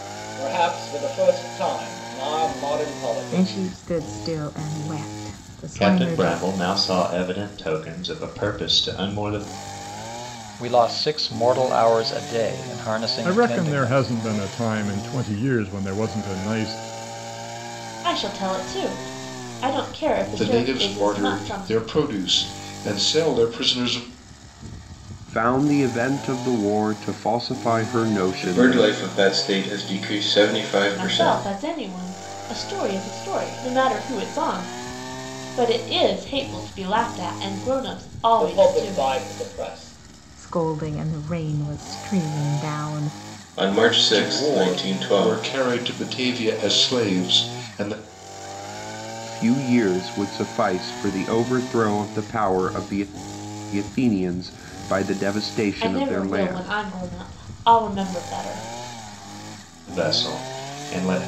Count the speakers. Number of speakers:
nine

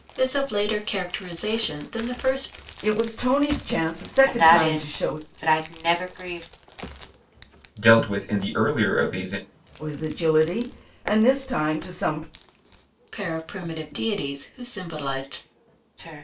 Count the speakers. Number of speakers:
four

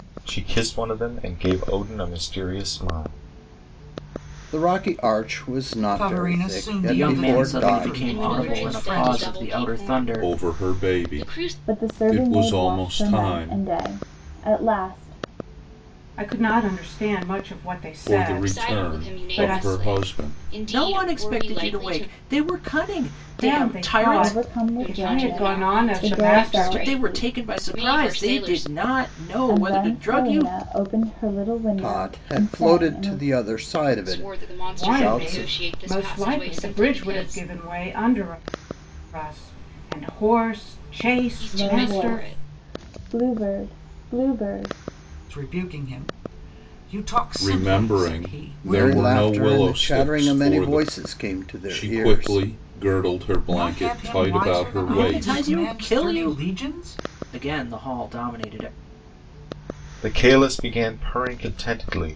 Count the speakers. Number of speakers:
eight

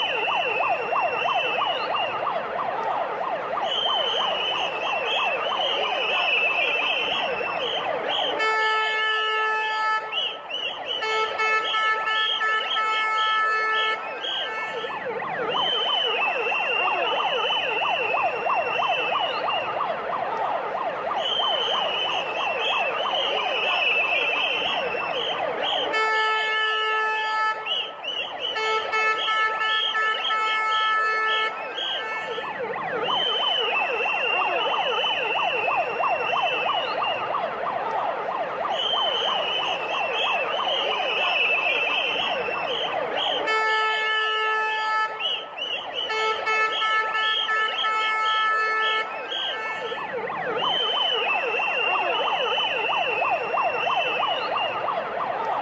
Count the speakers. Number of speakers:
zero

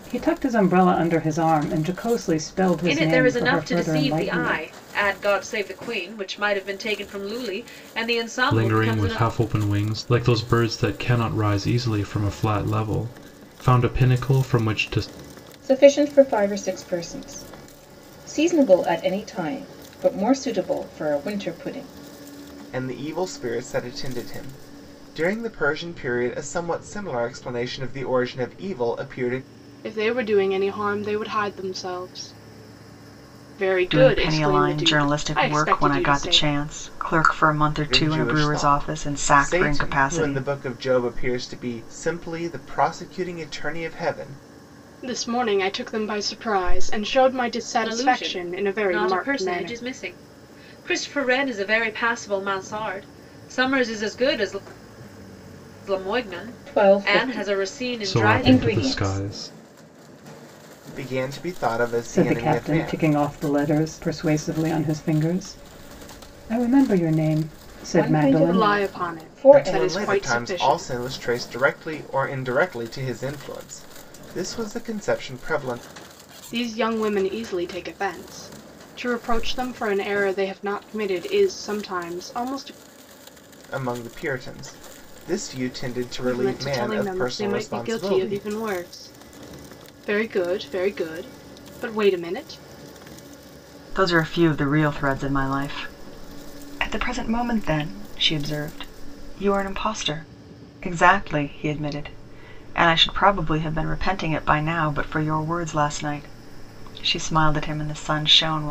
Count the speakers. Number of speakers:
seven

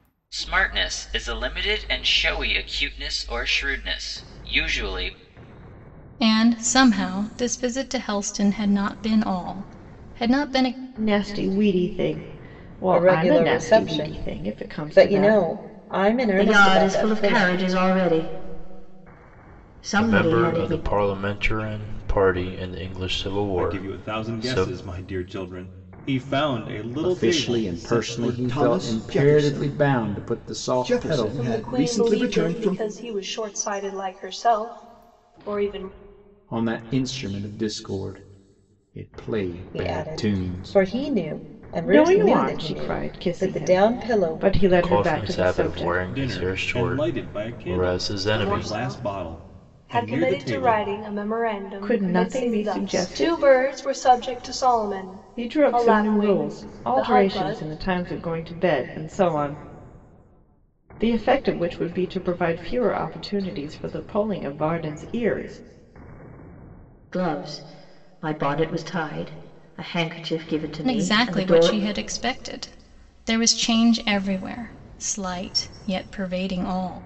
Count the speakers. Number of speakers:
ten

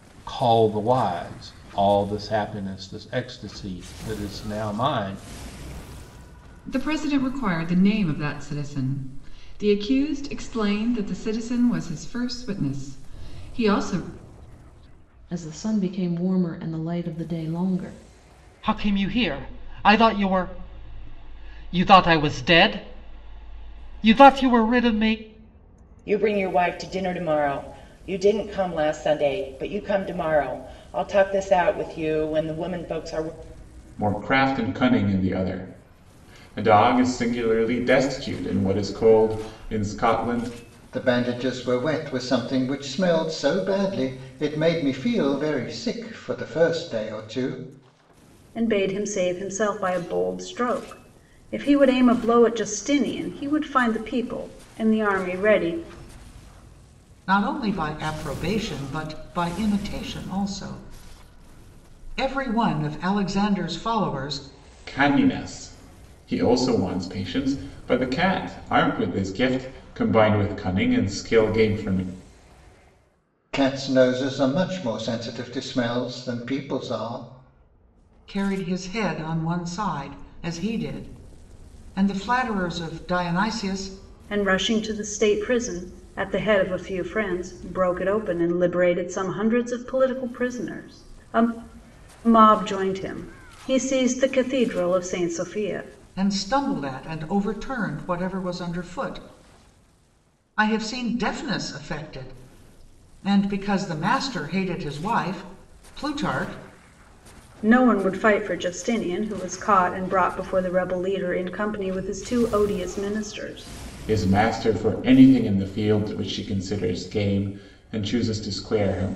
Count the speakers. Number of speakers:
nine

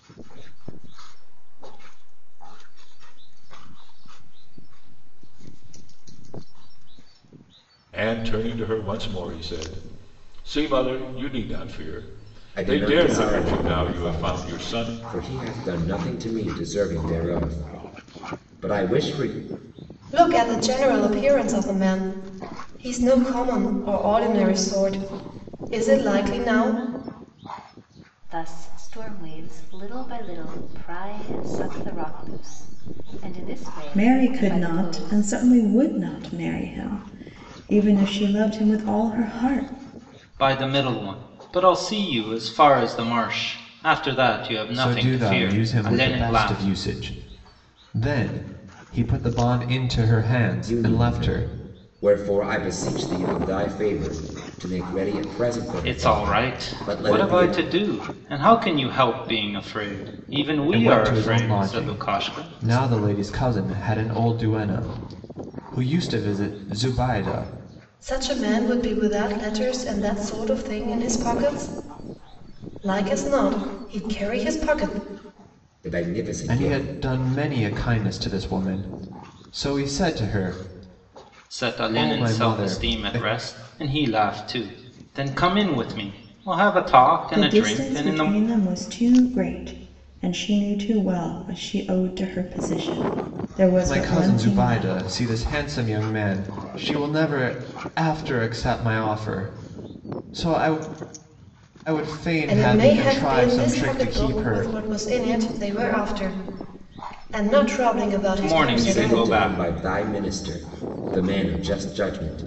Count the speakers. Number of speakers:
eight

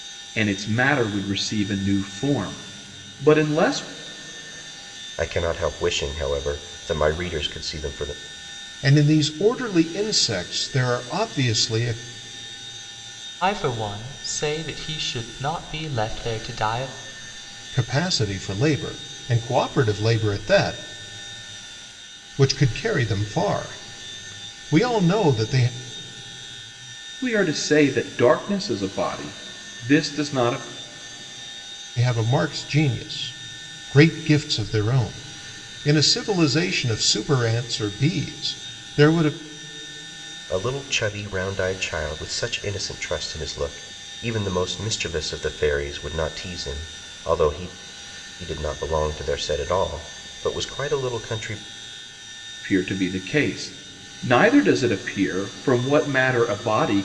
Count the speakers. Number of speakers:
four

